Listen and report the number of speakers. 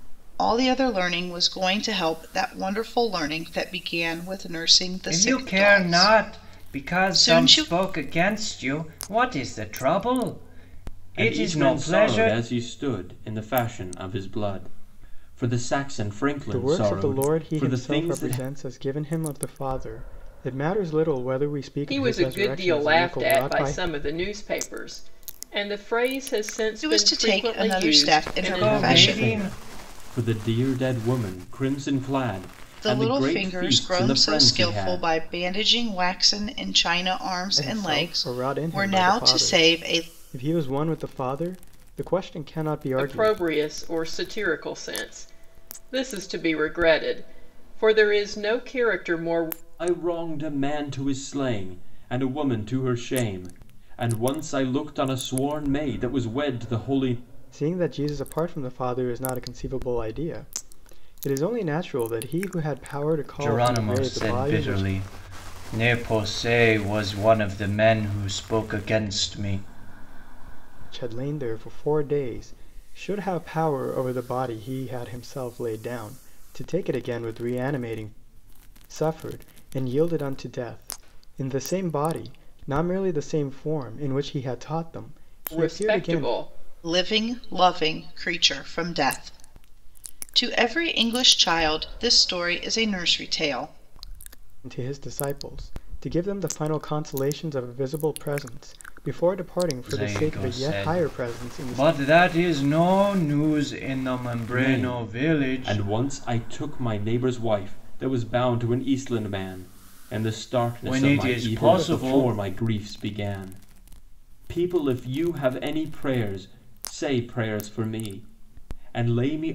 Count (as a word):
five